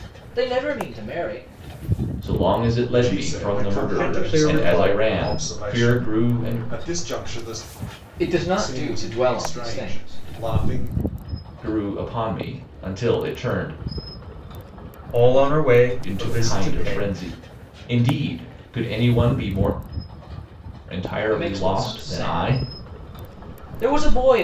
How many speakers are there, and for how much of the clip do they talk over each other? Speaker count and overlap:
4, about 32%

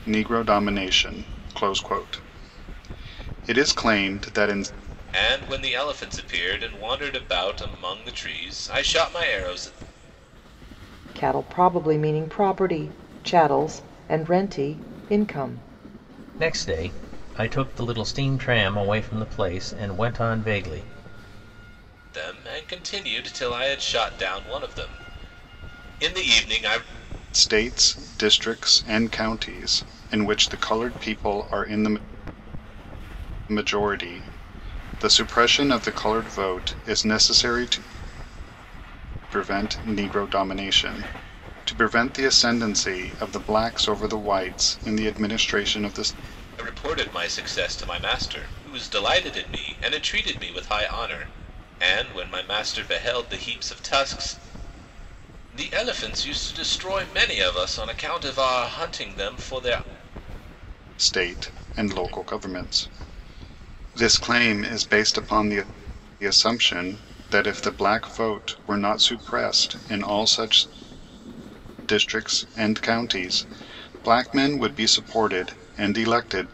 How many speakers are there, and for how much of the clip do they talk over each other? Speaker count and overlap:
4, no overlap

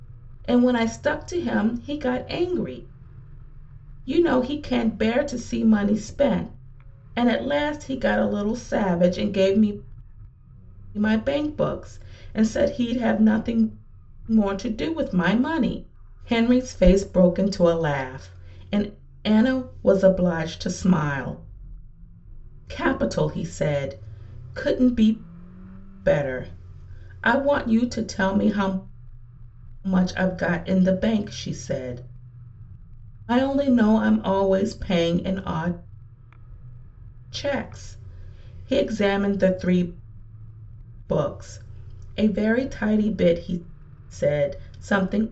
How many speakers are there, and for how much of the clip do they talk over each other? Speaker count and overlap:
1, no overlap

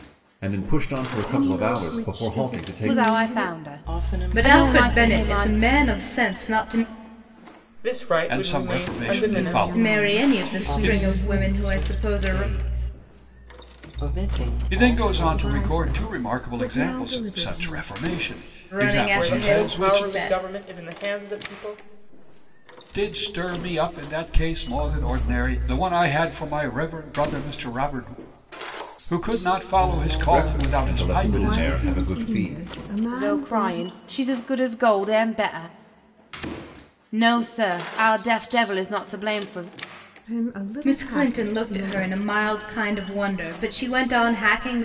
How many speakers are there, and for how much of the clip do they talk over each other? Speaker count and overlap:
7, about 44%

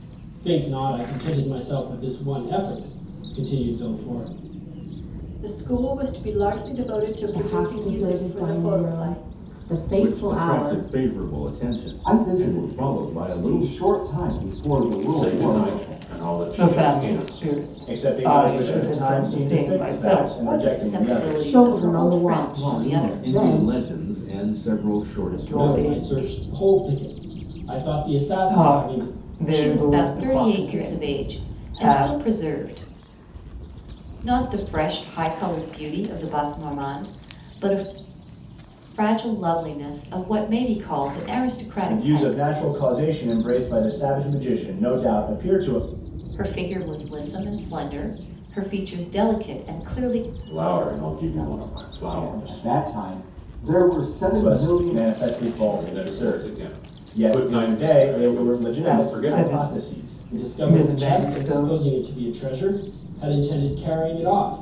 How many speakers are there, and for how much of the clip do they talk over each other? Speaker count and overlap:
9, about 40%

